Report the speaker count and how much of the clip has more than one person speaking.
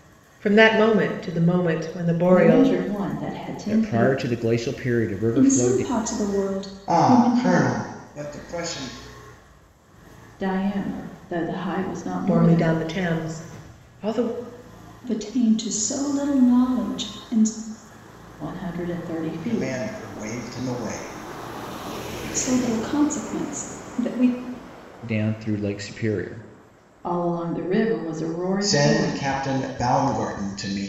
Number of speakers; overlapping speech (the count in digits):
5, about 13%